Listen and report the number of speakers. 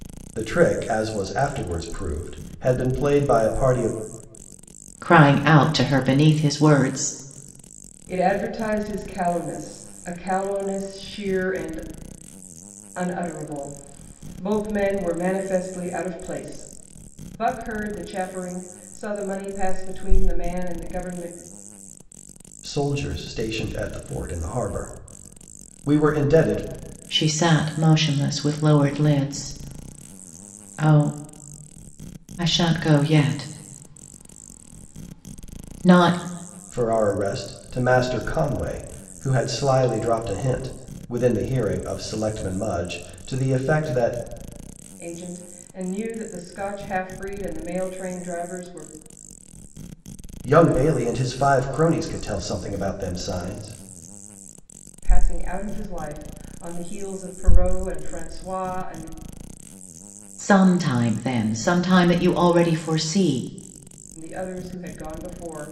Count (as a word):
three